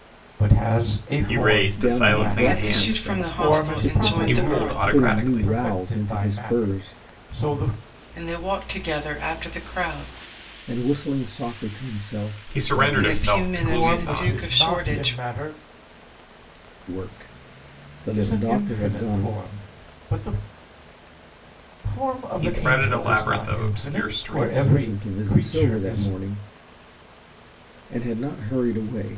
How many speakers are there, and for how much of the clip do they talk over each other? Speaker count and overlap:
four, about 46%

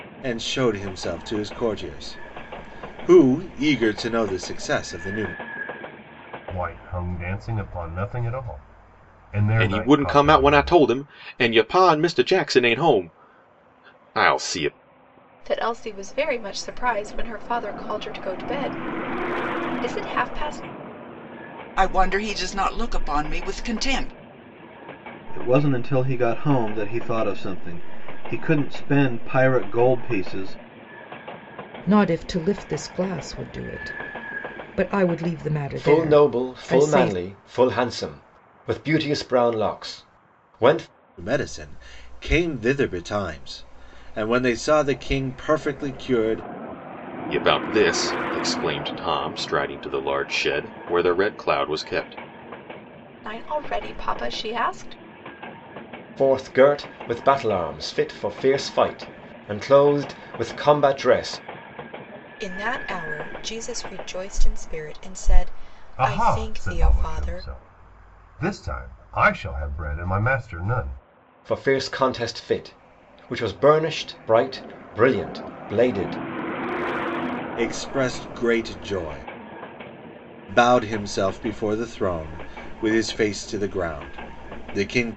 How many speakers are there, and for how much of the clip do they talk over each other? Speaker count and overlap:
eight, about 5%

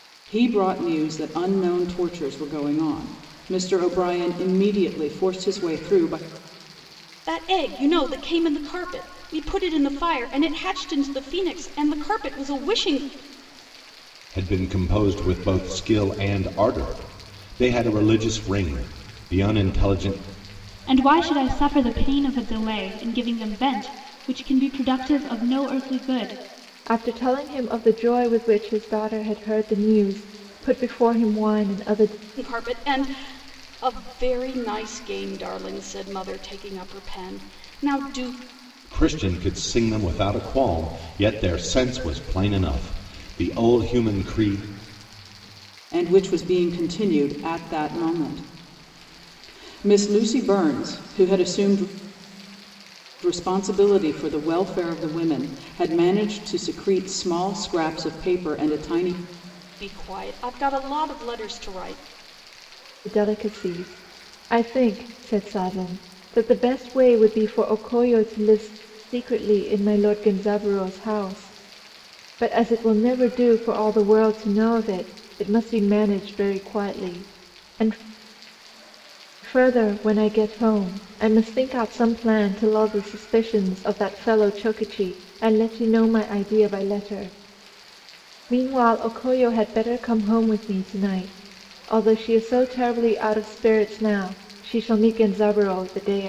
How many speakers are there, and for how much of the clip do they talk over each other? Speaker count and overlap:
five, no overlap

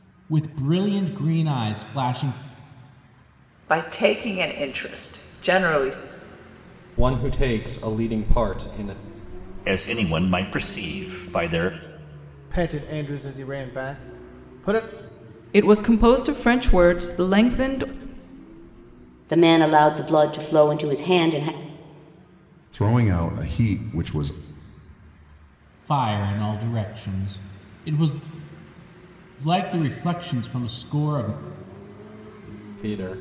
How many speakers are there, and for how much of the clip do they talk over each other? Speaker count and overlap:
eight, no overlap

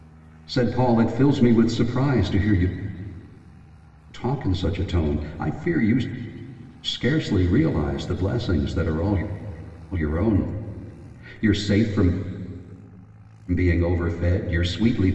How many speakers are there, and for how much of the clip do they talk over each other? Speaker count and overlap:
one, no overlap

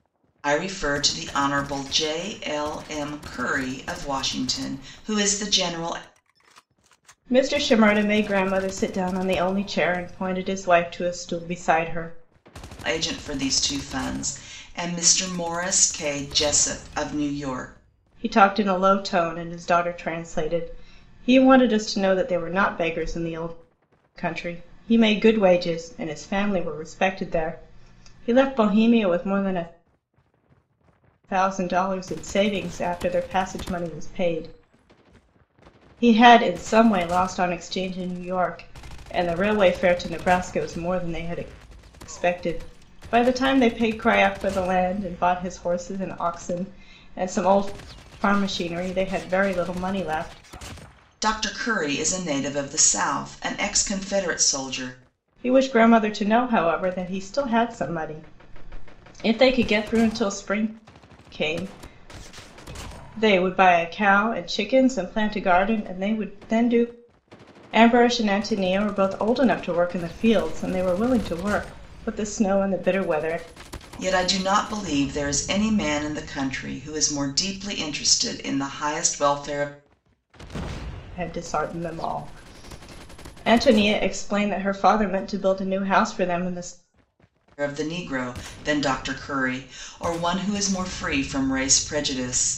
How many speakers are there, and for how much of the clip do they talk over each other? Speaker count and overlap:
two, no overlap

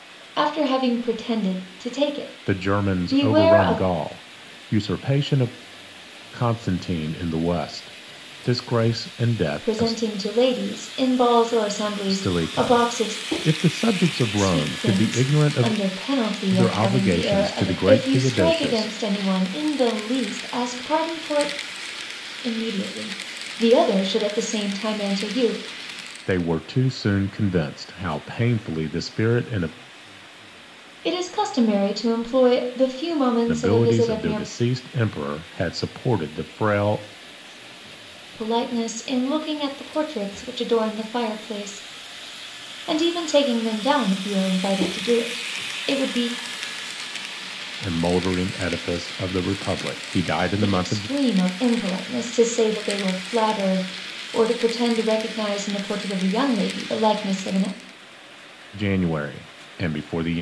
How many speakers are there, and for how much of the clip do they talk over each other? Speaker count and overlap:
two, about 14%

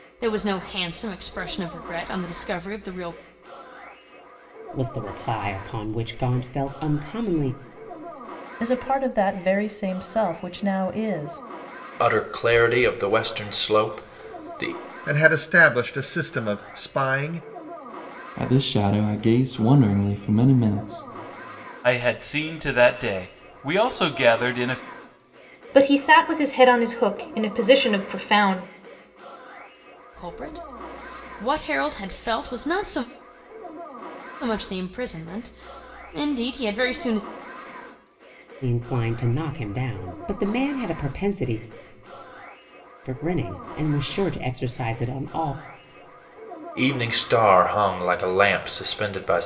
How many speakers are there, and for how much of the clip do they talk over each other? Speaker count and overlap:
eight, no overlap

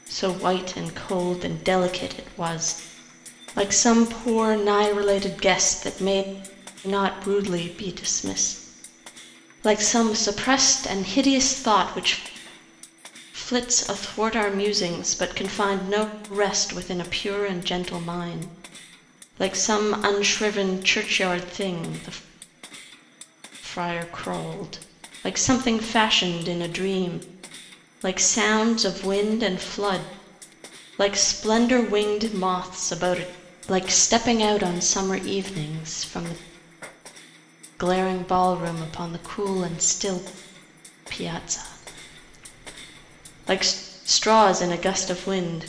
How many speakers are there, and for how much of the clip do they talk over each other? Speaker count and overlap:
one, no overlap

